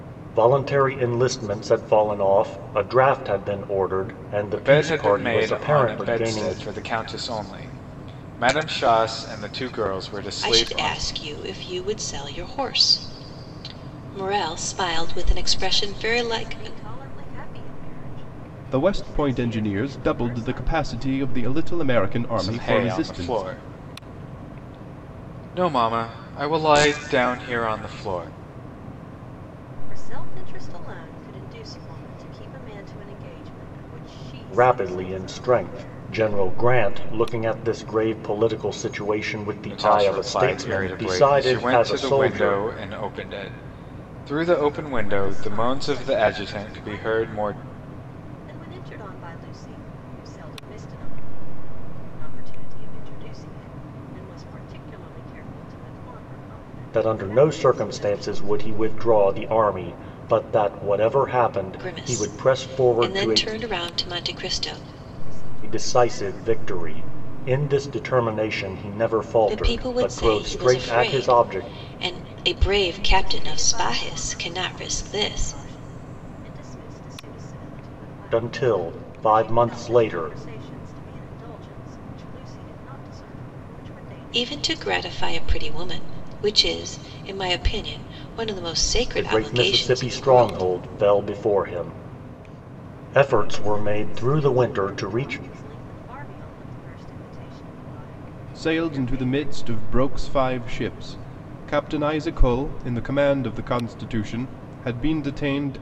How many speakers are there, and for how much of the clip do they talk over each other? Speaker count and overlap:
5, about 31%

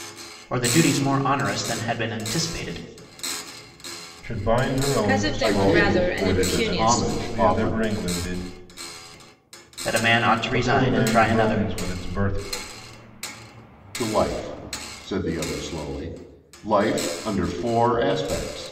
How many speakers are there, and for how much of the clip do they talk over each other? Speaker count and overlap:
4, about 22%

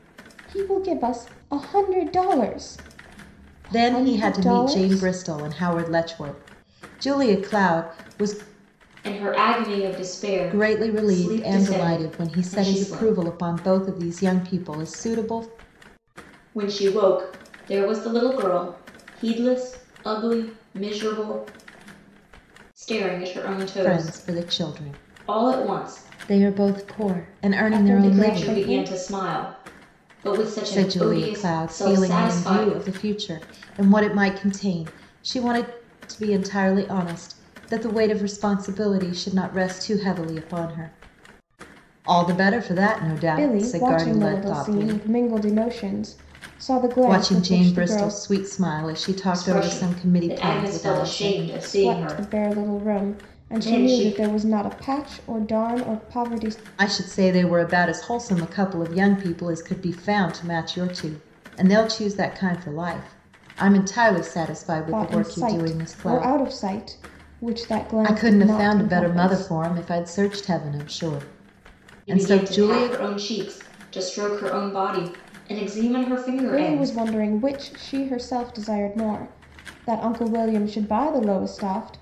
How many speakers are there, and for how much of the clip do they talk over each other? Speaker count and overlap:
3, about 27%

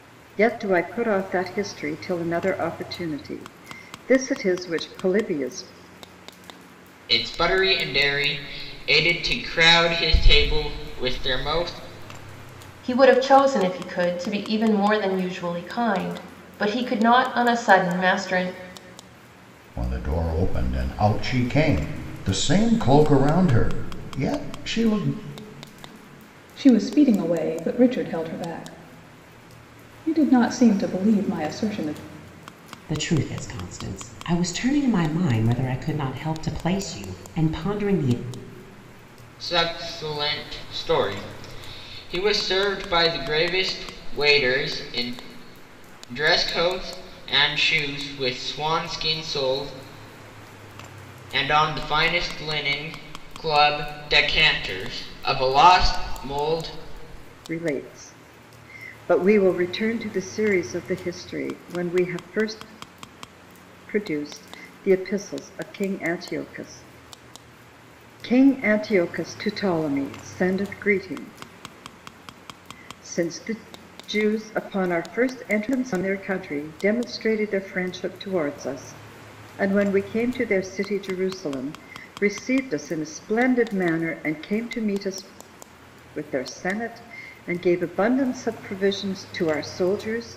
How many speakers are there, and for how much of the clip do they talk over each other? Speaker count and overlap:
6, no overlap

